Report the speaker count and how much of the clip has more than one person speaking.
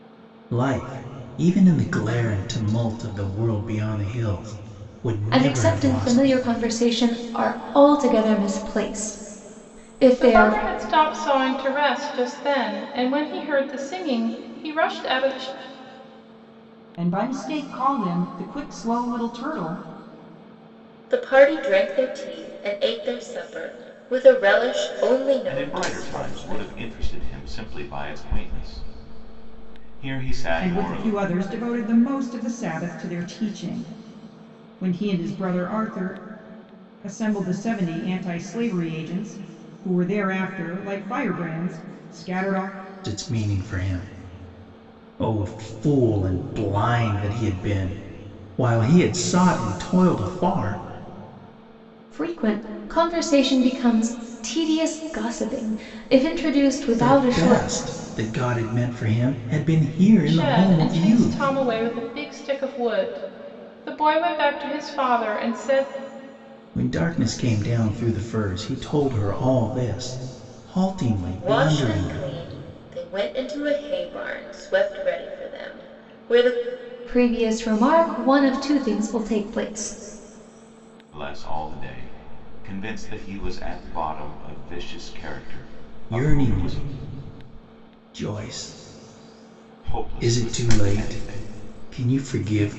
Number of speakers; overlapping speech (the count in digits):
6, about 9%